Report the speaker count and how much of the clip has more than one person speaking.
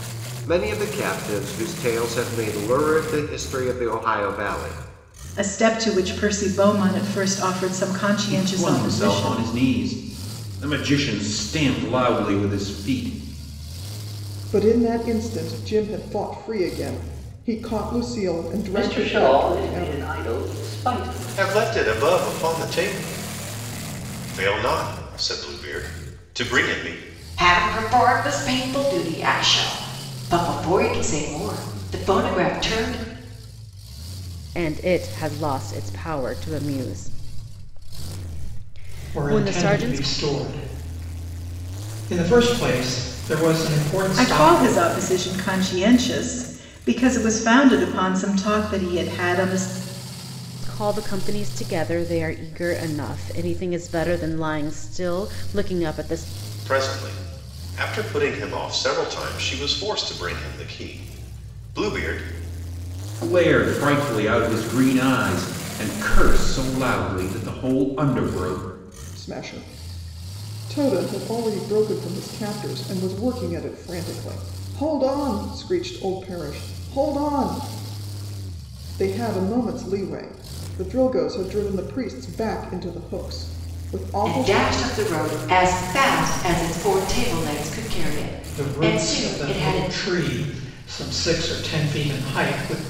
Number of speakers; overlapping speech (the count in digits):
9, about 7%